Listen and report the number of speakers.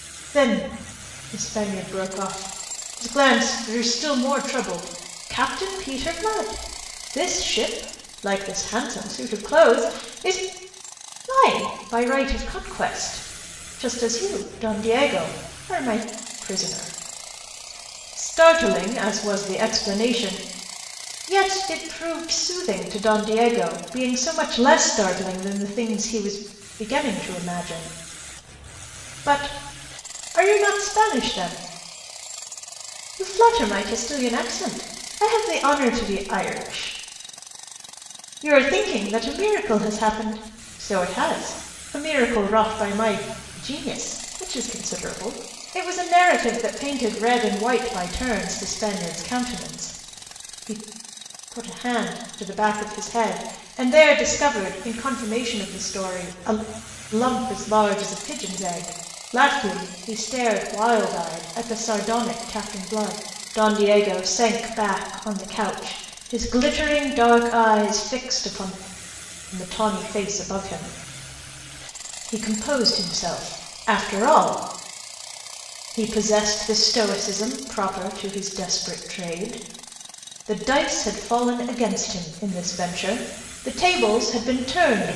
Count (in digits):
1